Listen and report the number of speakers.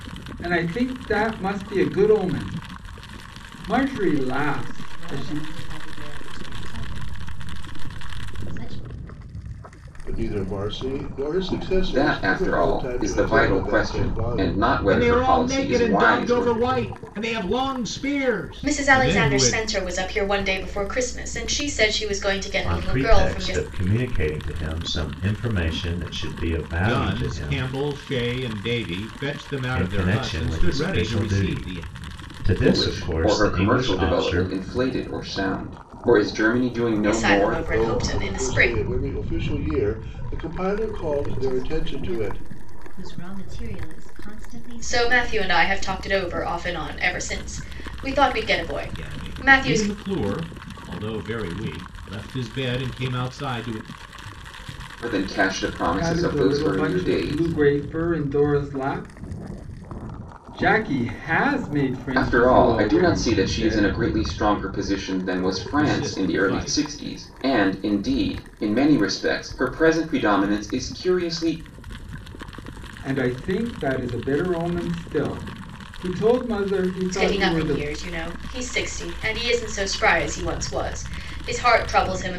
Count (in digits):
7